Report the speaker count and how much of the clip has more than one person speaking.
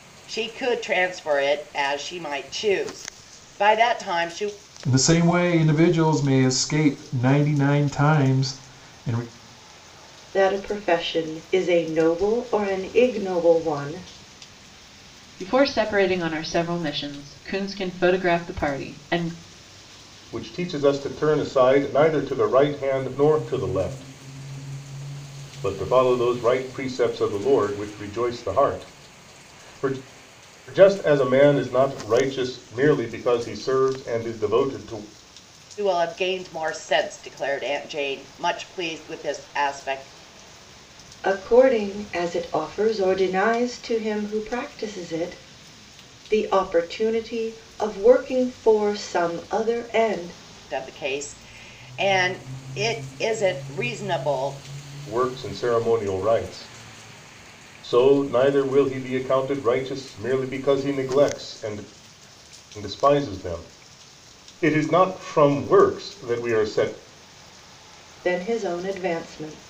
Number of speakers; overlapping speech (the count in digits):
5, no overlap